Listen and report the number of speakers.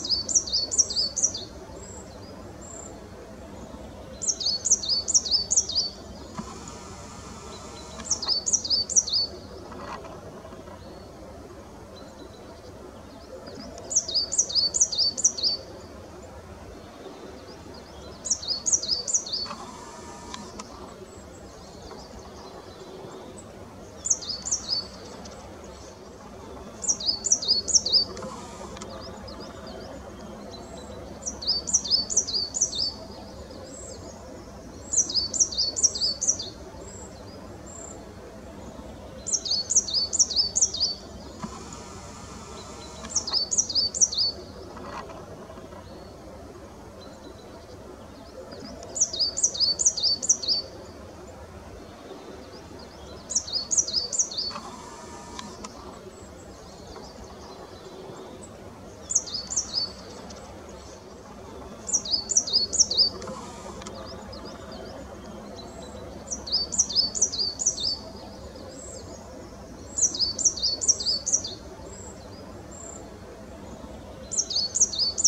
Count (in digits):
0